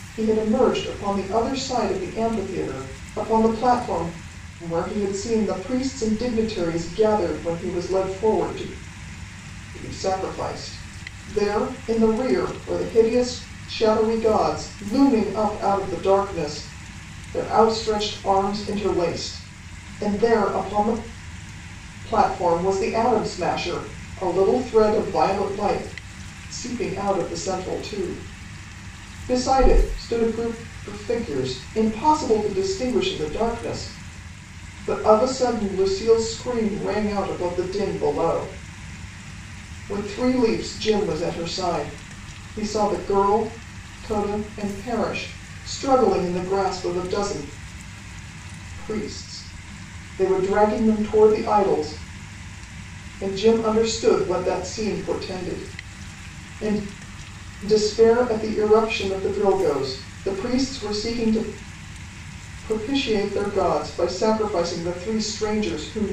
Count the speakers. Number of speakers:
1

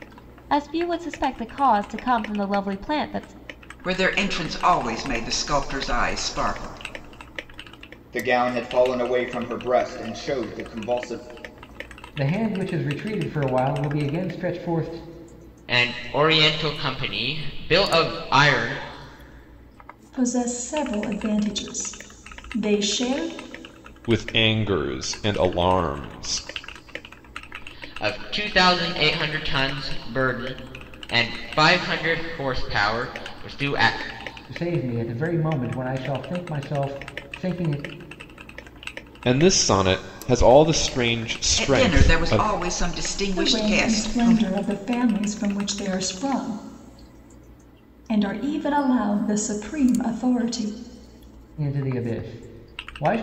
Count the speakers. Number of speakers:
7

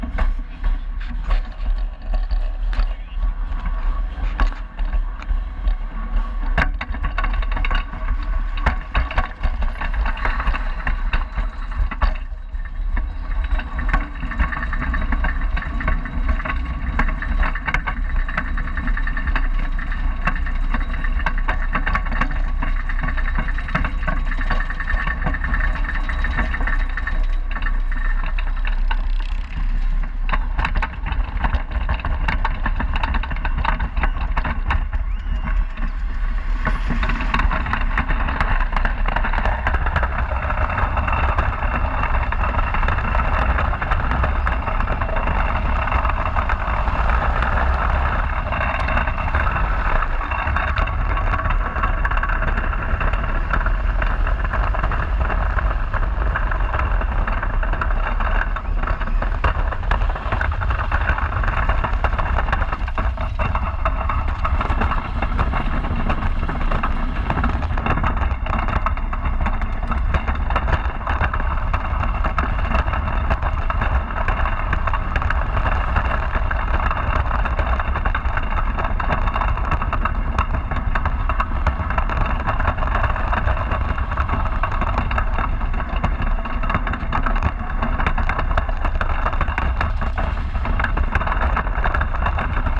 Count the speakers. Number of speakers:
0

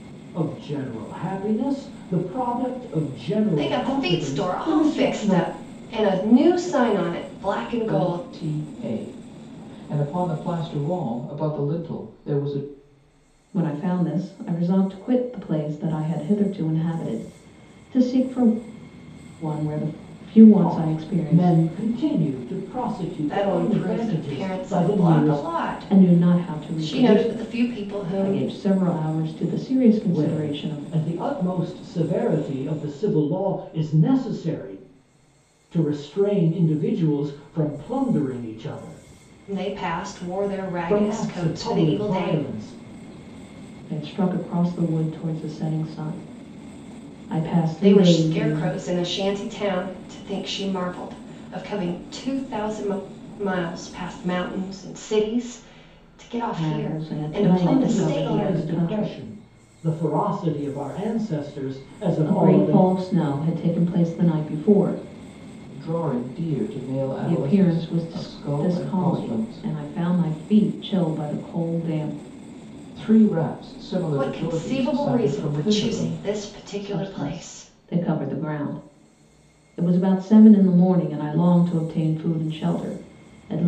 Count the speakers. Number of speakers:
4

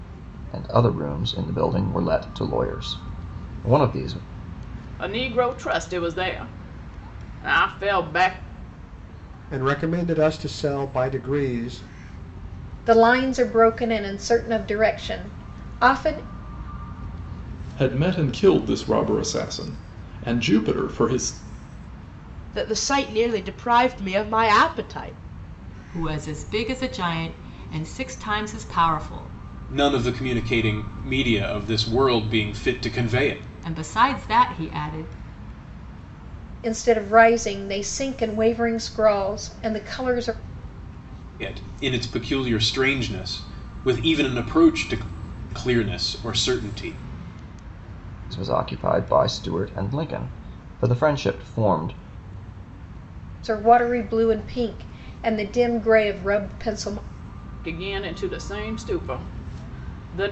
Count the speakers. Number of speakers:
8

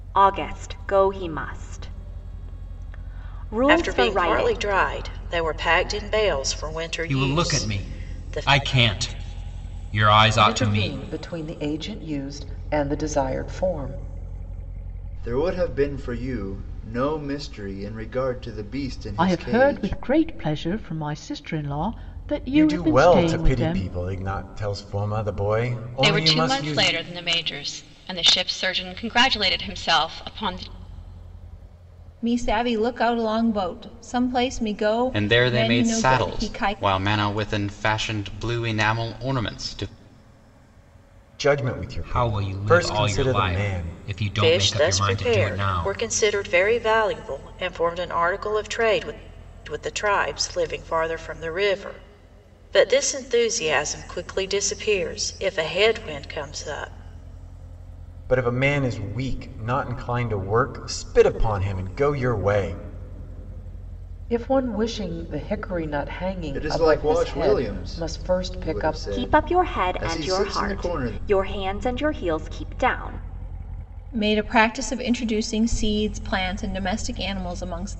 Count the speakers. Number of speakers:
10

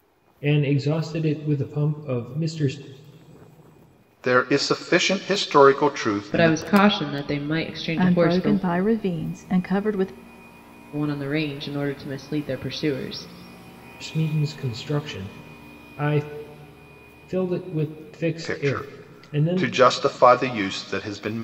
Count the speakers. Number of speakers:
4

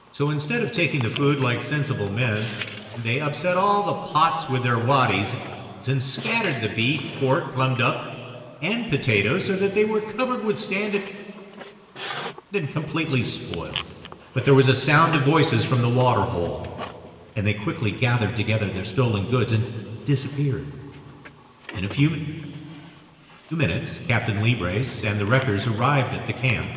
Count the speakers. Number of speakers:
1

